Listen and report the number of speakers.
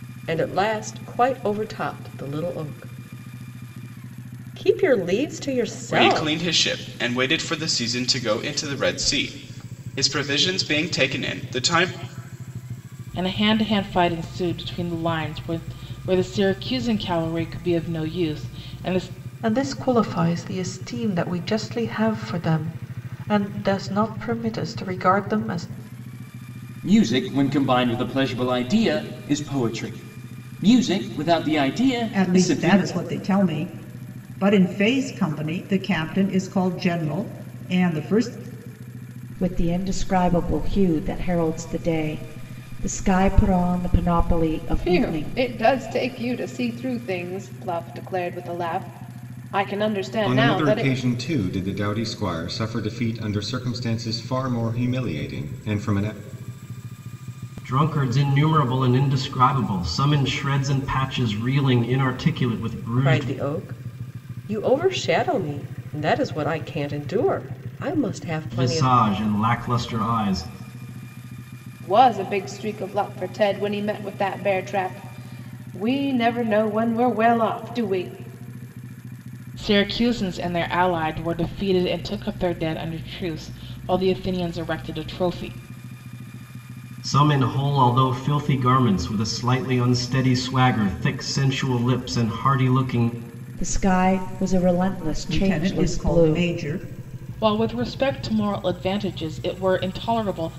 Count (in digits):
10